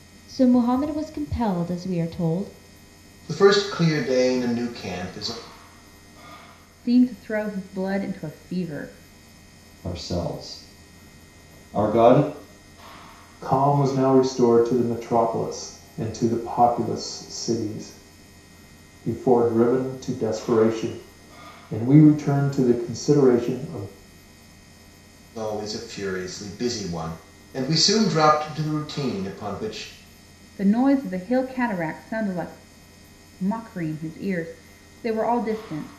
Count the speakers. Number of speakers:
5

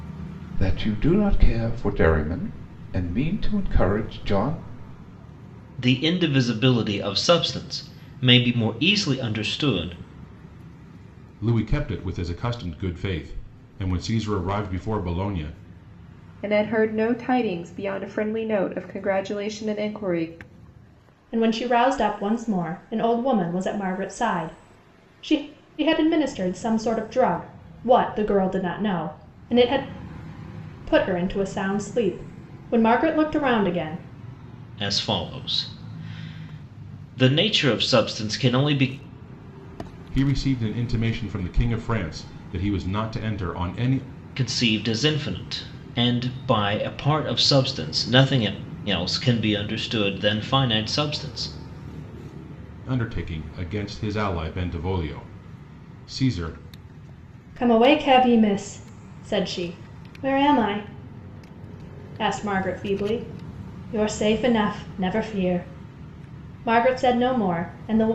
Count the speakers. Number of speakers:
5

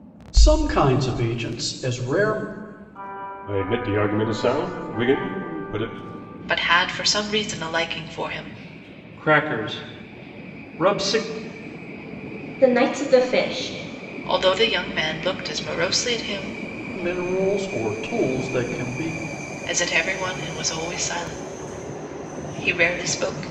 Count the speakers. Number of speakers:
5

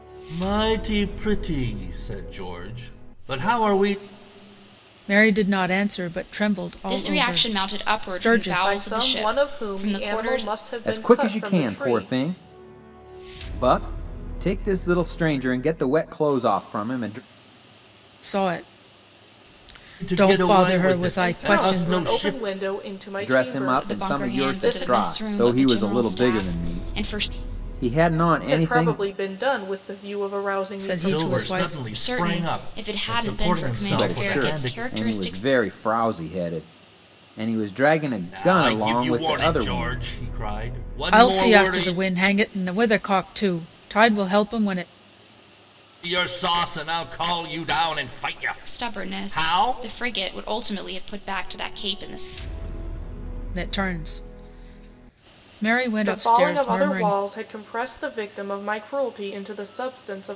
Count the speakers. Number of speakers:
5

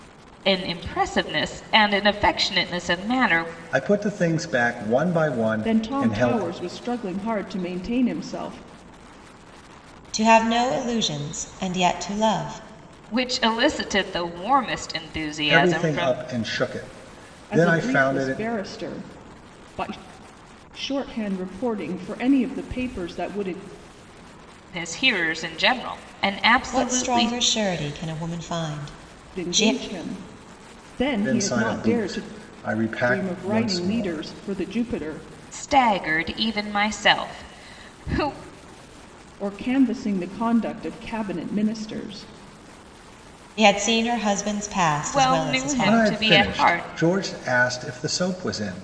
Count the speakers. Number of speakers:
4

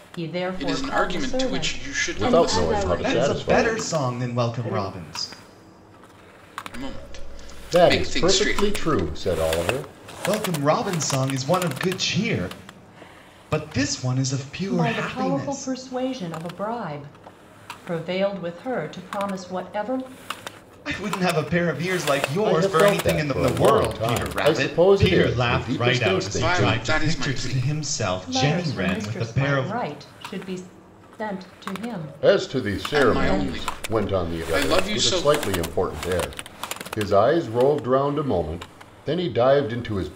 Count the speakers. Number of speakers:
5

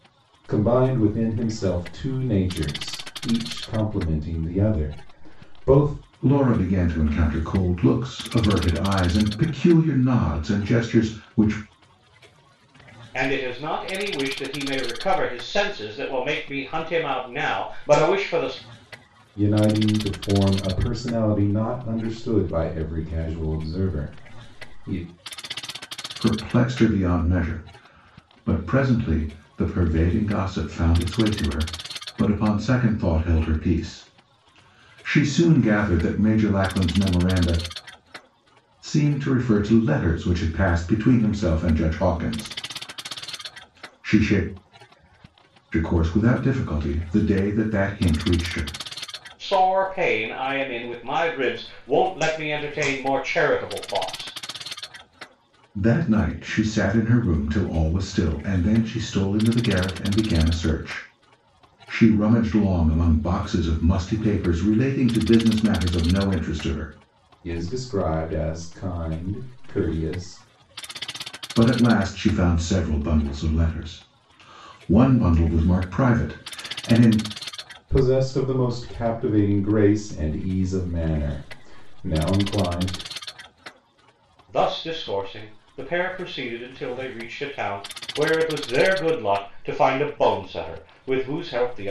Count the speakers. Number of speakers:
3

